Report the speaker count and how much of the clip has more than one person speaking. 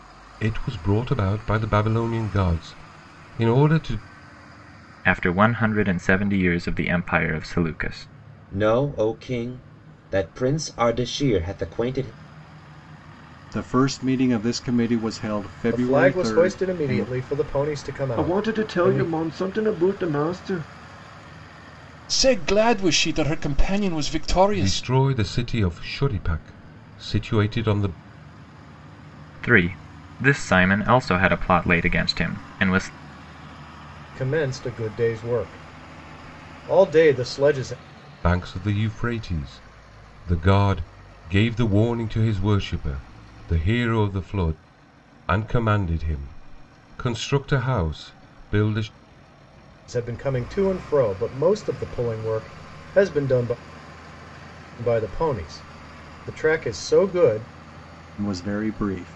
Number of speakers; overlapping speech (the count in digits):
7, about 5%